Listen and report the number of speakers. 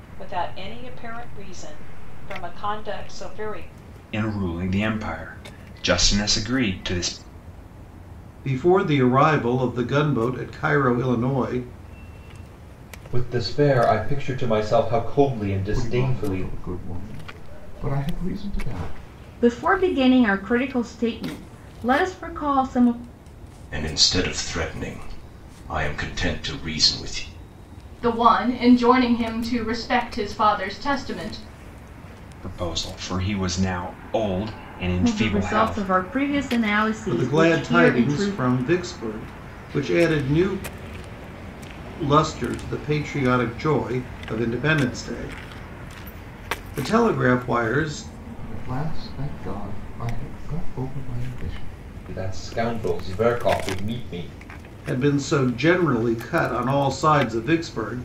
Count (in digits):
8